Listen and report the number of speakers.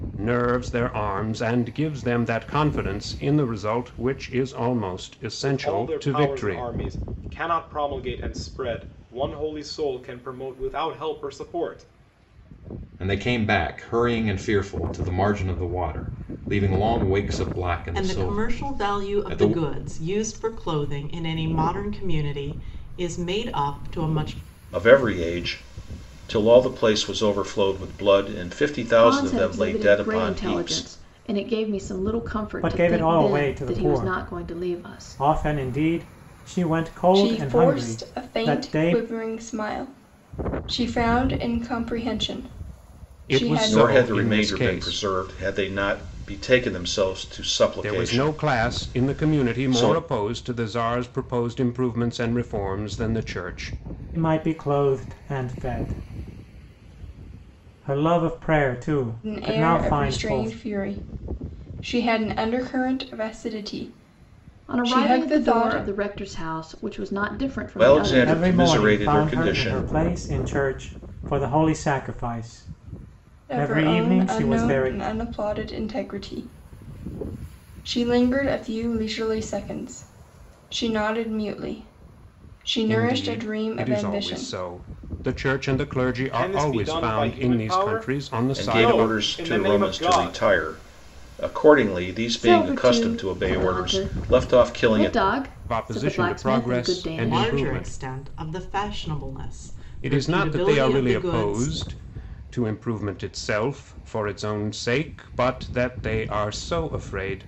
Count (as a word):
eight